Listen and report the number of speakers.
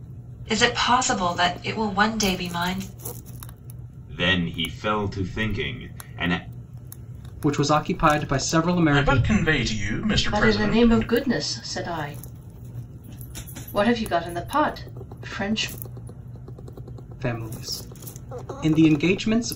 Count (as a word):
five